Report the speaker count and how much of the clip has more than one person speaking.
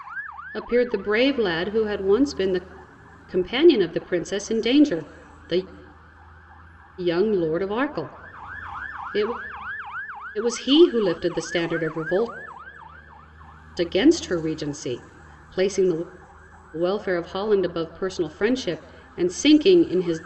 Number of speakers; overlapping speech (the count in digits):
1, no overlap